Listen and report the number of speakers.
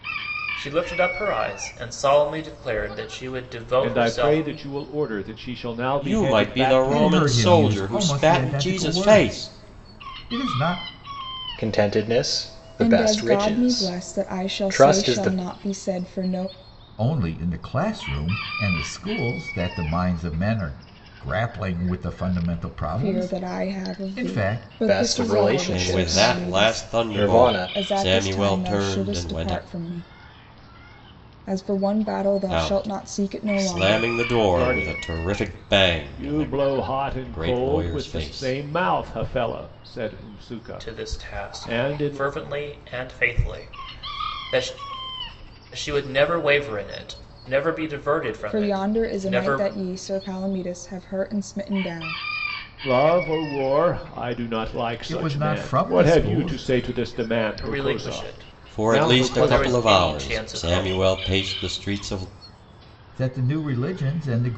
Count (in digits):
6